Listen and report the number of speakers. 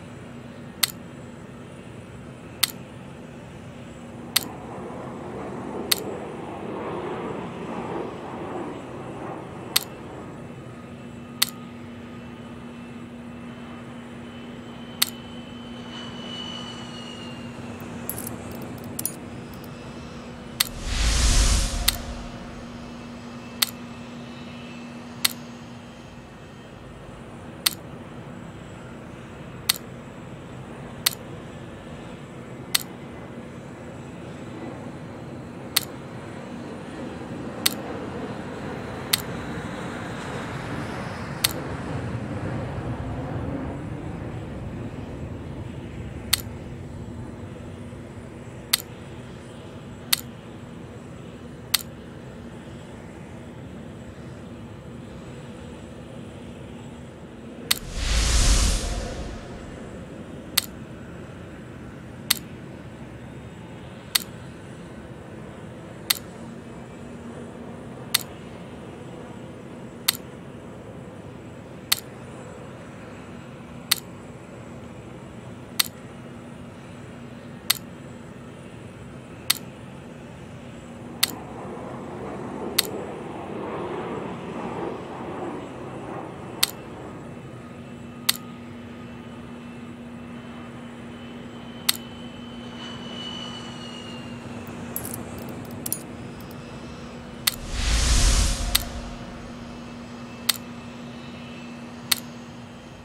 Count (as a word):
zero